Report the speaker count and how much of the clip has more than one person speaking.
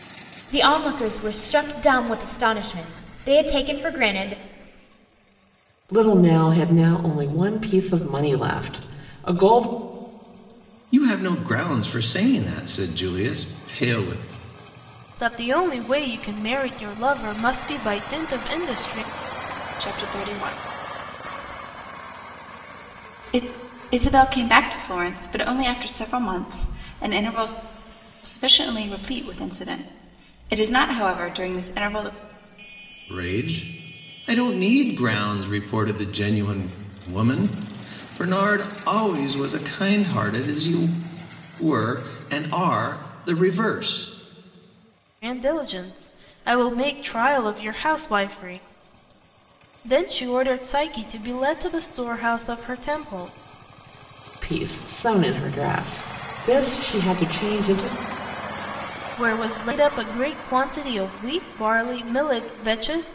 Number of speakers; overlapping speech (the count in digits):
5, no overlap